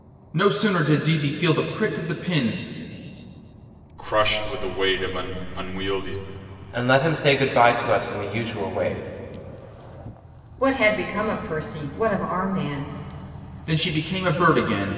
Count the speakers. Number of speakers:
4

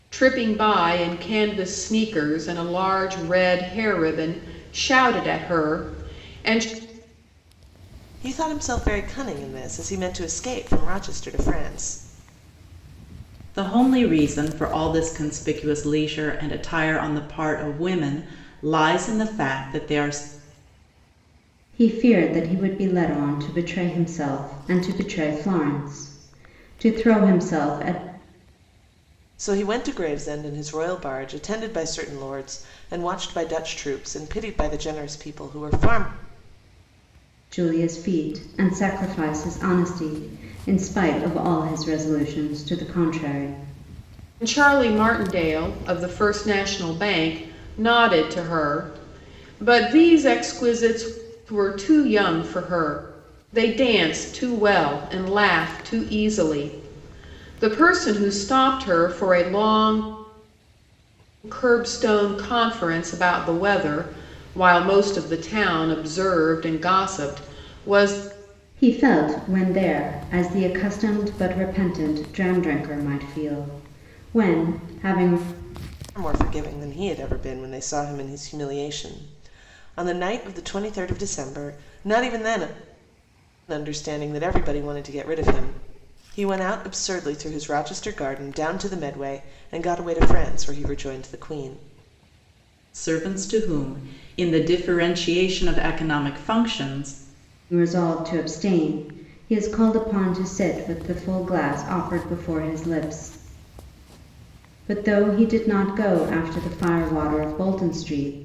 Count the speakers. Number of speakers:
4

